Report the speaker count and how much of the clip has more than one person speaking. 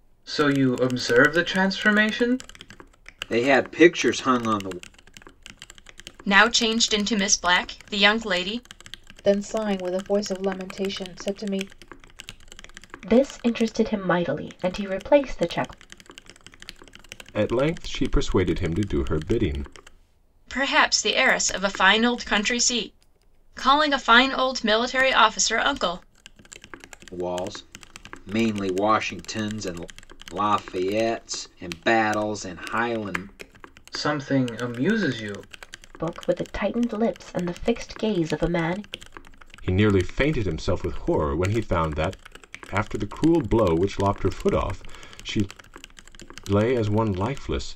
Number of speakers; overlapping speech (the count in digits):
6, no overlap